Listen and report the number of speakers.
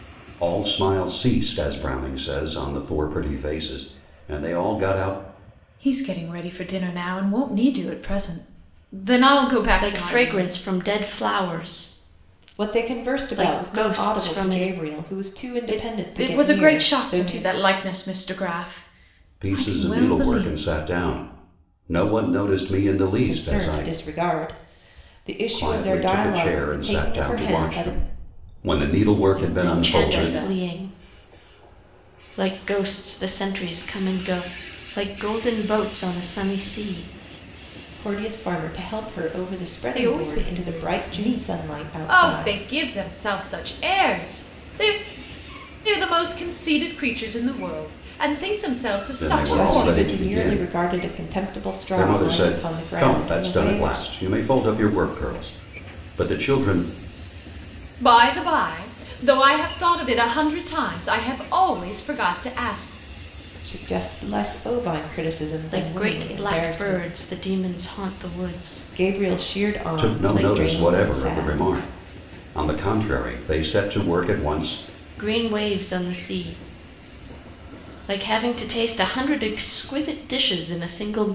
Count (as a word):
four